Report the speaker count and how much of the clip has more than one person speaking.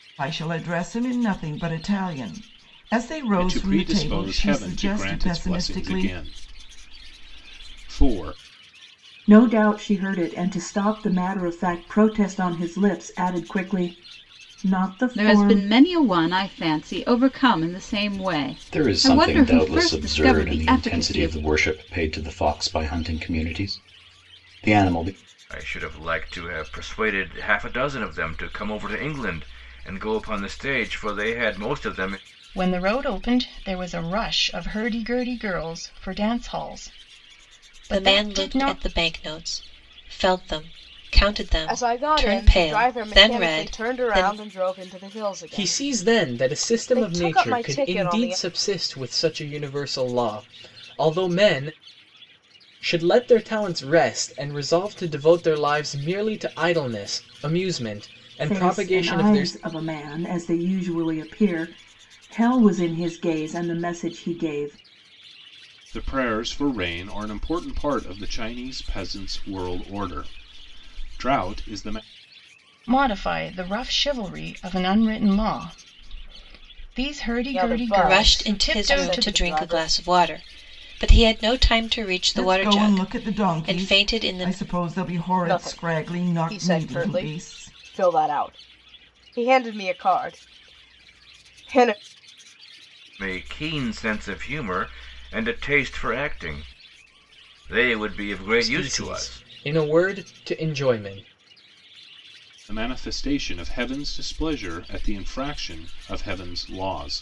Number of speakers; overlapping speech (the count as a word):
ten, about 20%